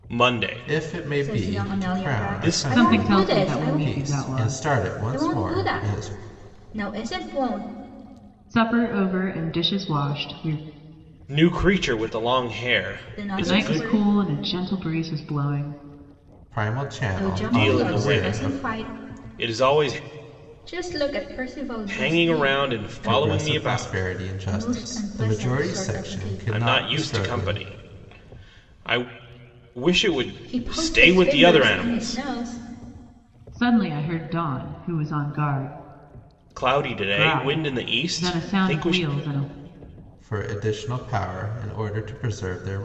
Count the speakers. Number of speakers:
4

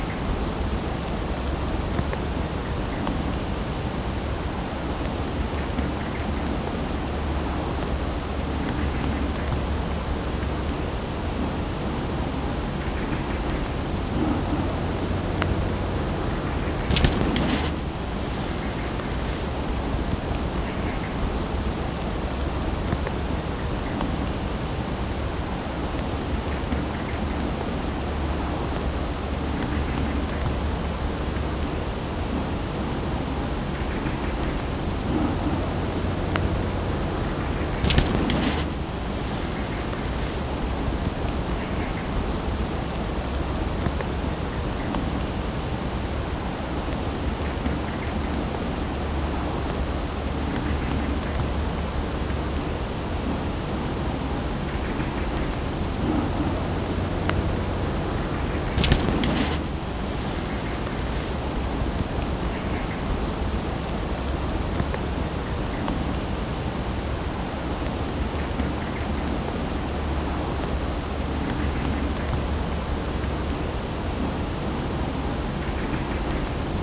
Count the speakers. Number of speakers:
0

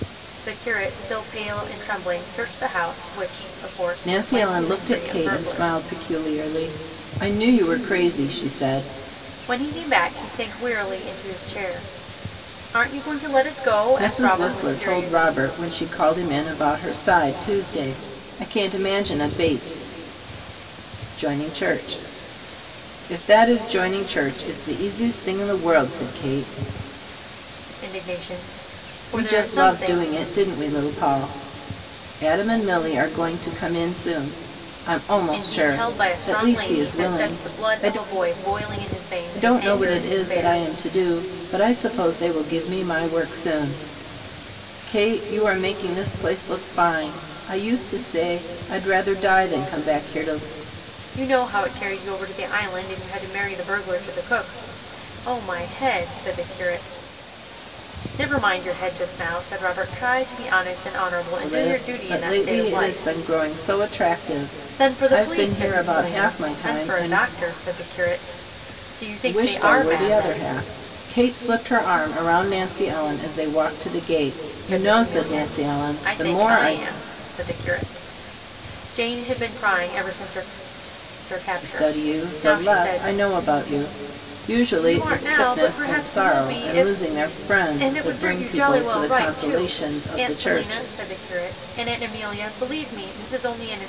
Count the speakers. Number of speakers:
2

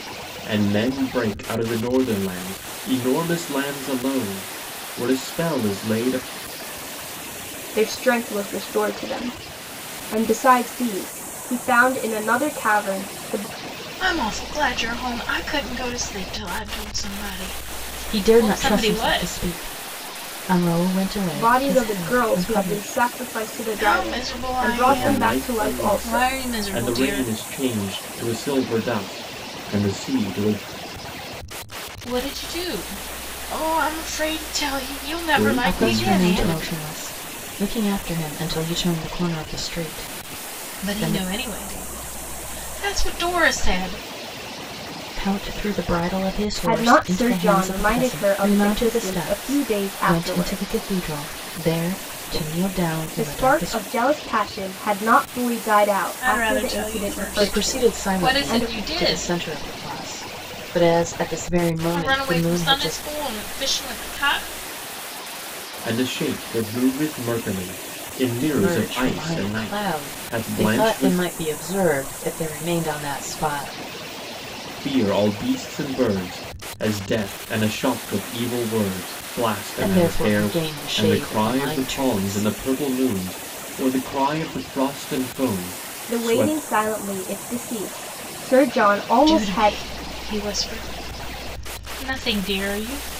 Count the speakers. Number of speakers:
4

